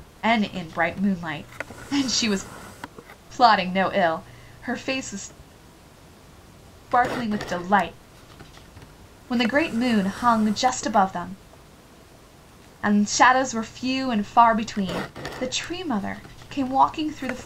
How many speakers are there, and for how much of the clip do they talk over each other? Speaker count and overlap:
one, no overlap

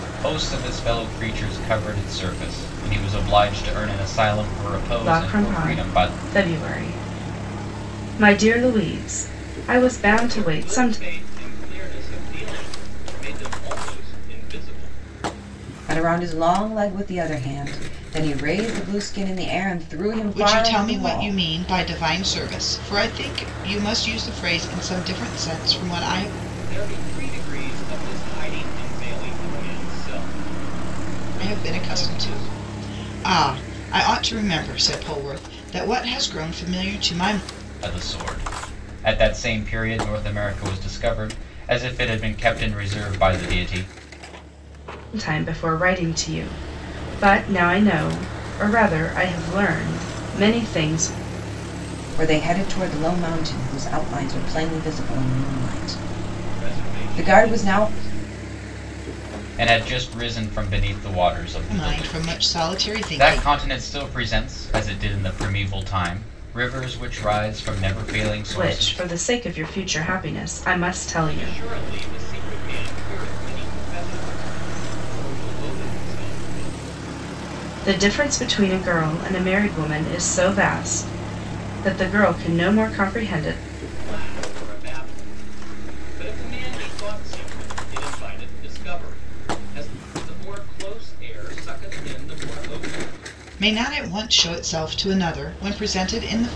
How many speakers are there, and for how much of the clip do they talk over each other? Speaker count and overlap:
five, about 8%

